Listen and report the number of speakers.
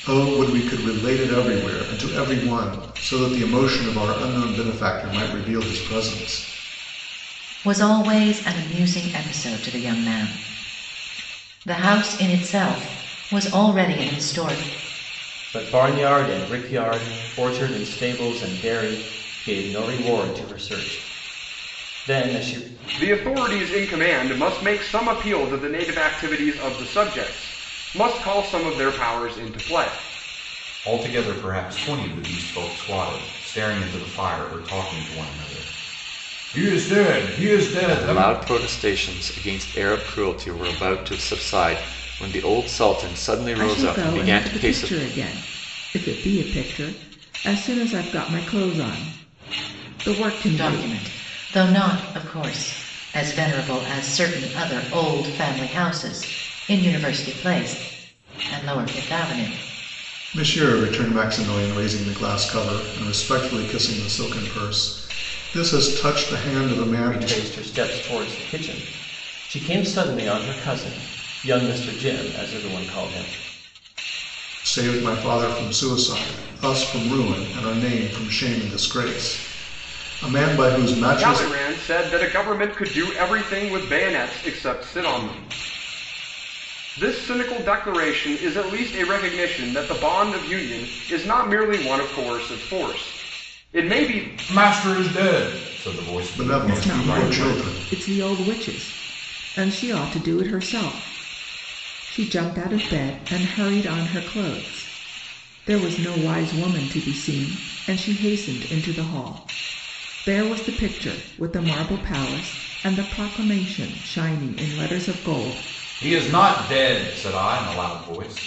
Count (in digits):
7